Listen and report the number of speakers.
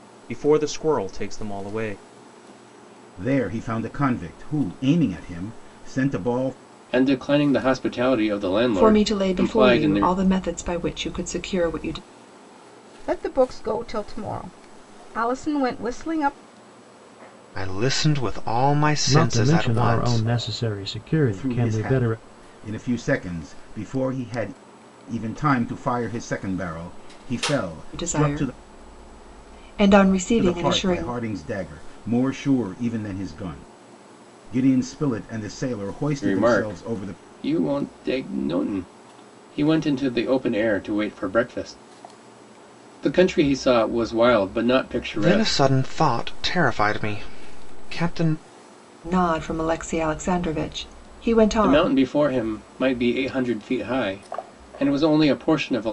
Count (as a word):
seven